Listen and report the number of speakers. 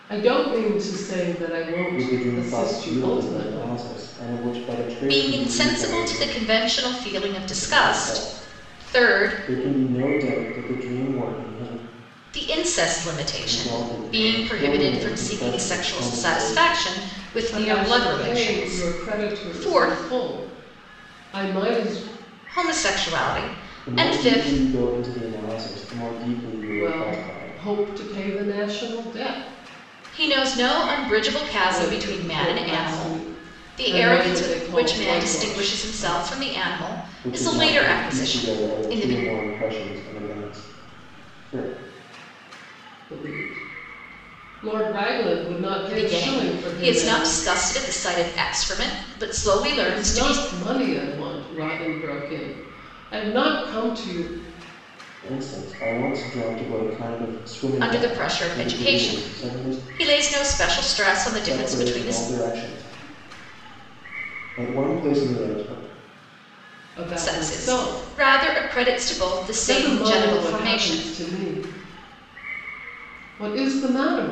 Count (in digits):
3